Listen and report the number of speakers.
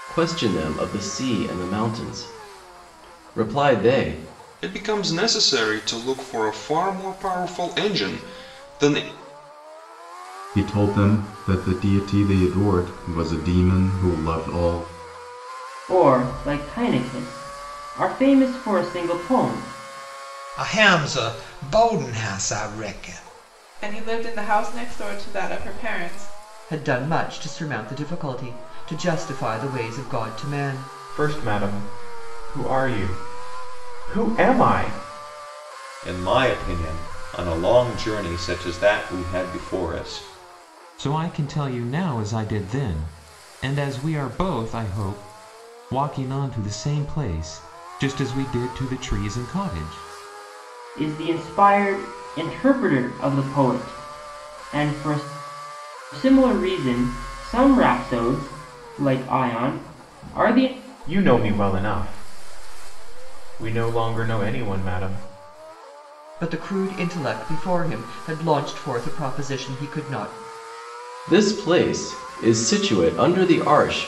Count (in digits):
10